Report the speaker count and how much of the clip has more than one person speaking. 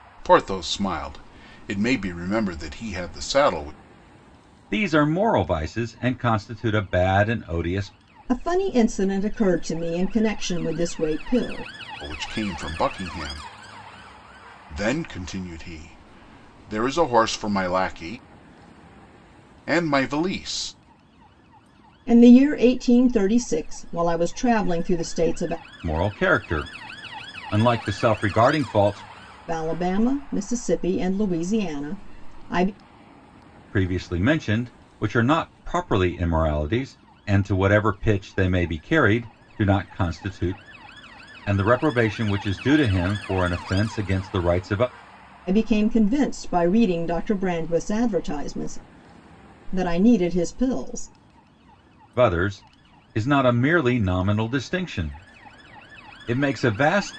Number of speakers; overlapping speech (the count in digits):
3, no overlap